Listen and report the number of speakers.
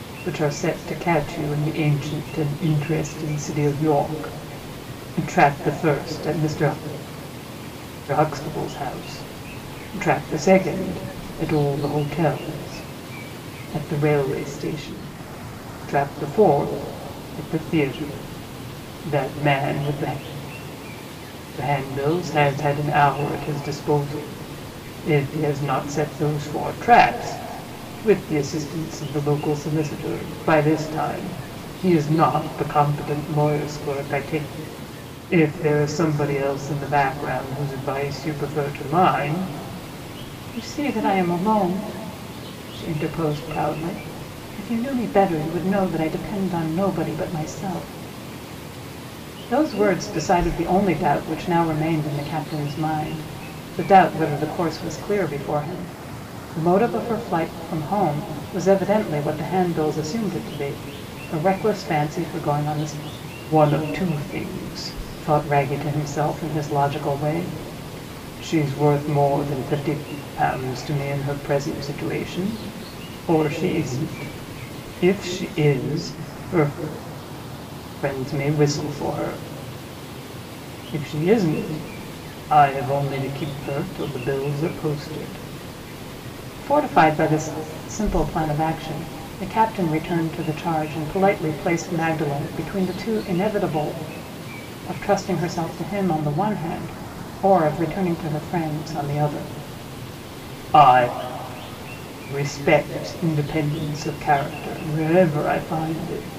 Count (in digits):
1